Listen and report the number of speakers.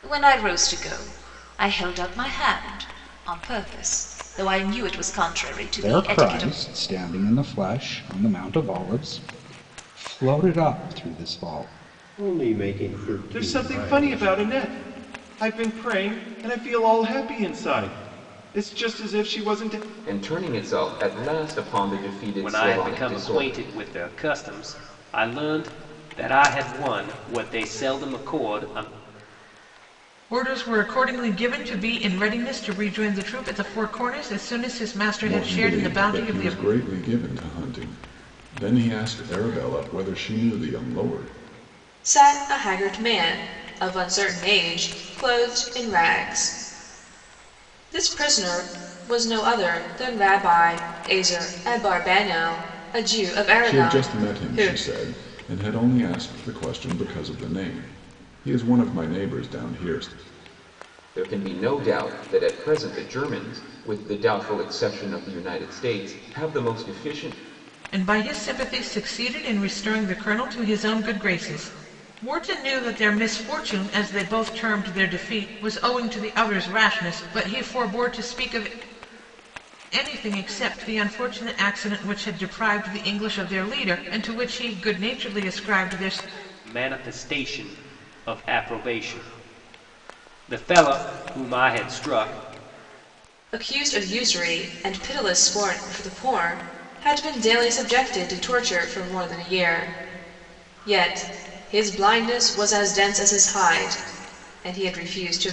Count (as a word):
nine